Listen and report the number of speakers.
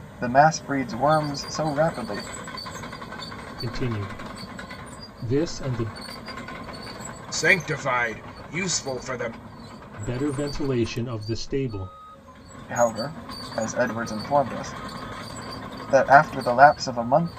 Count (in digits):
3